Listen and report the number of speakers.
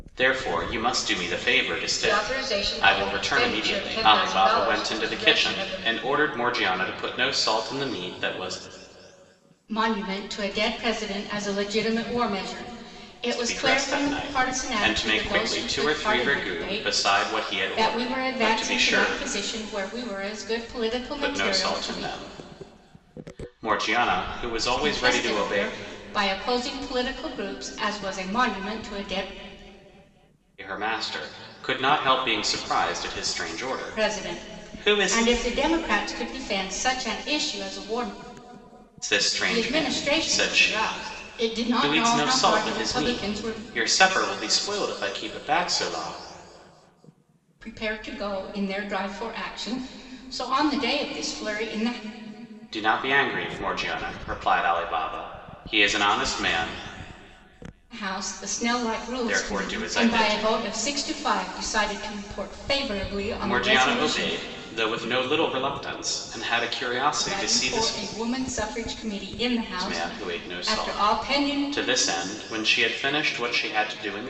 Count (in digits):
2